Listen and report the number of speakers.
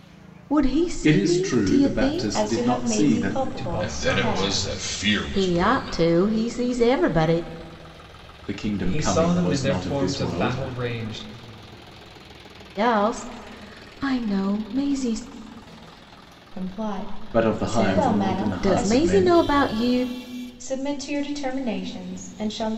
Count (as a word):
five